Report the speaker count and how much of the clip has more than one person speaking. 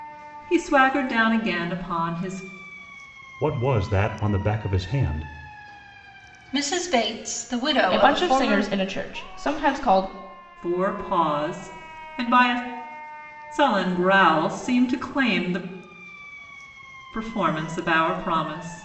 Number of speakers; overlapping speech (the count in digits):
4, about 4%